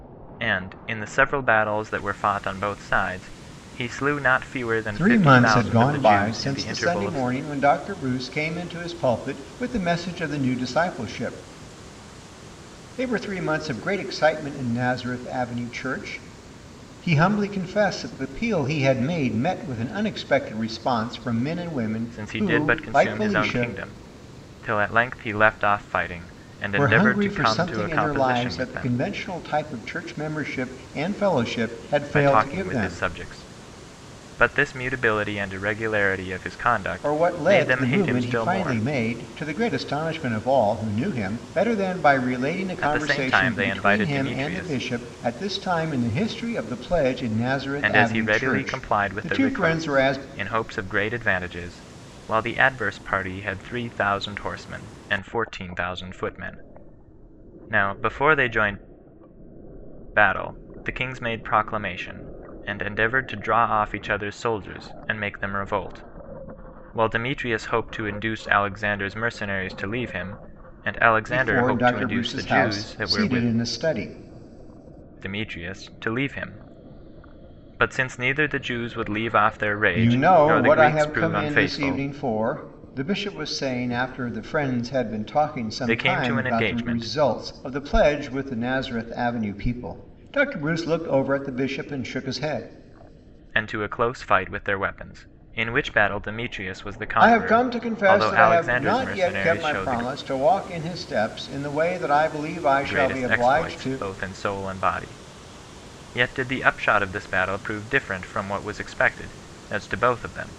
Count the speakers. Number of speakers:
2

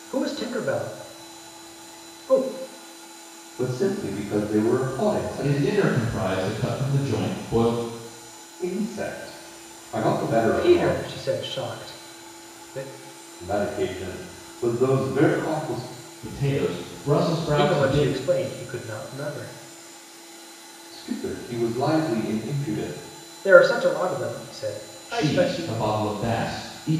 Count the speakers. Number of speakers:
3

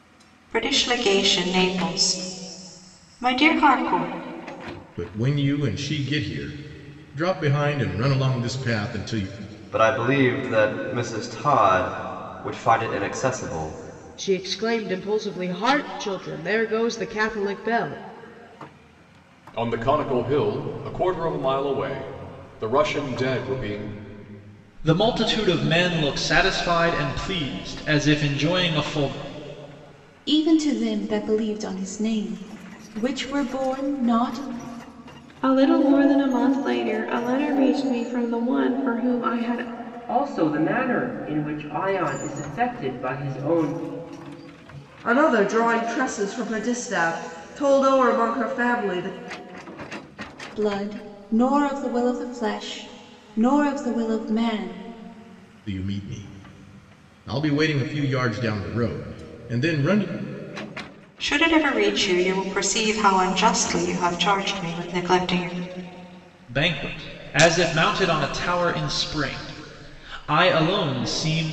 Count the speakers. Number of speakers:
10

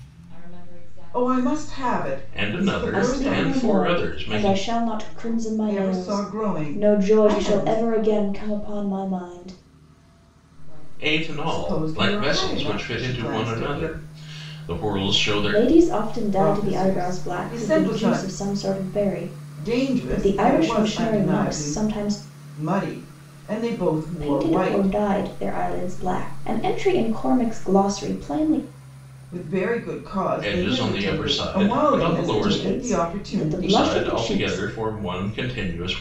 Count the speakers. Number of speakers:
4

